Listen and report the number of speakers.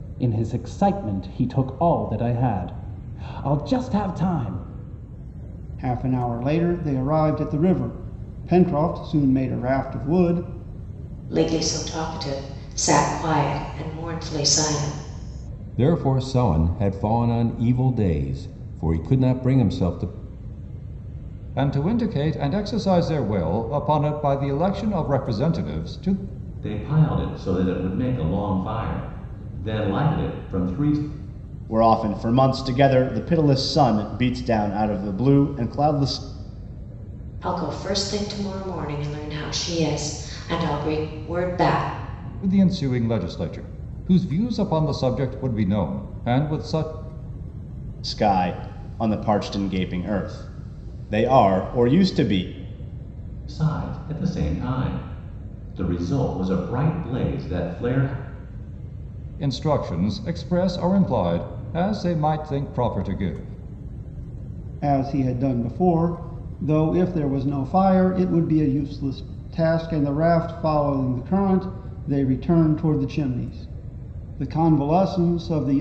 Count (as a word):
seven